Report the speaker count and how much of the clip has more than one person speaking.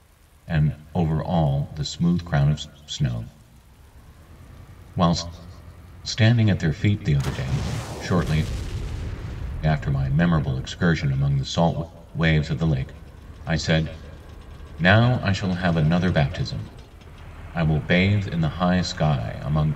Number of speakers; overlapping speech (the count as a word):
one, no overlap